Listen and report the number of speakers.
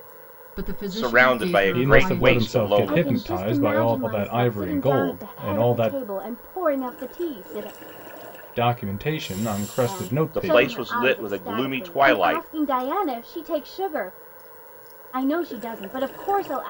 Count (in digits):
4